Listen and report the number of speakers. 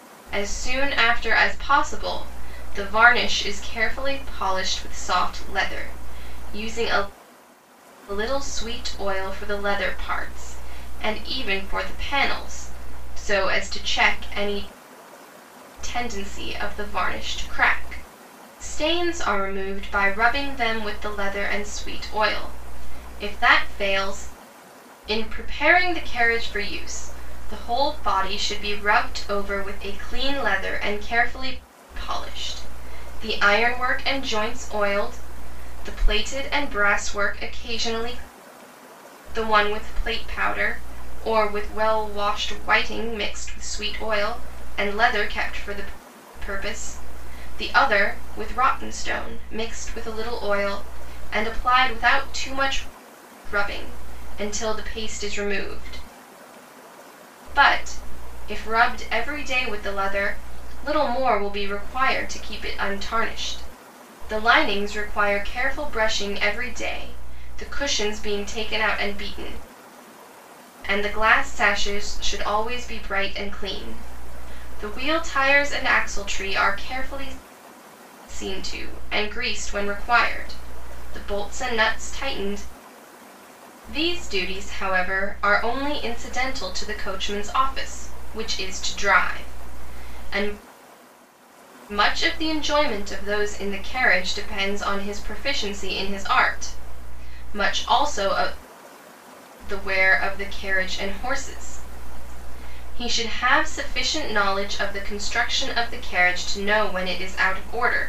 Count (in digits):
1